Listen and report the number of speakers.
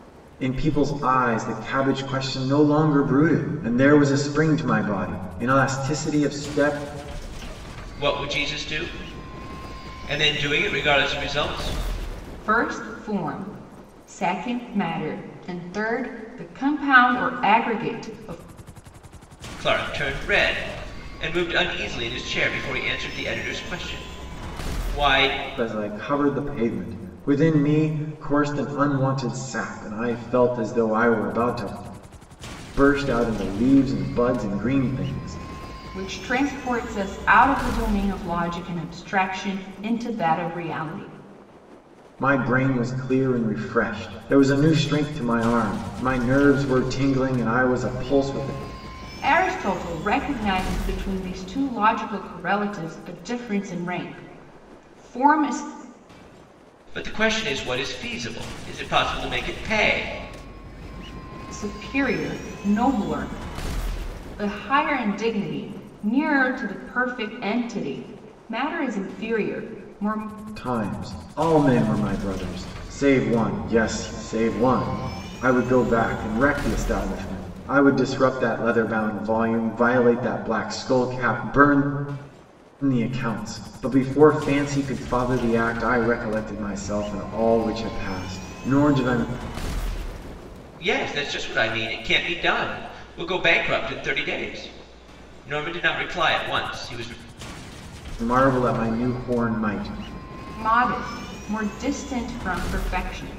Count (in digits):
3